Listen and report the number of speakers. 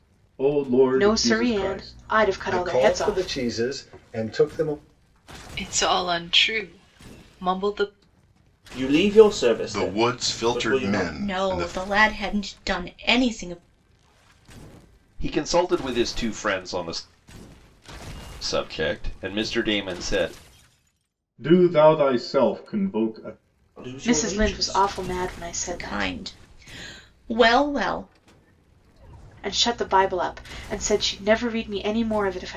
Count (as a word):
eight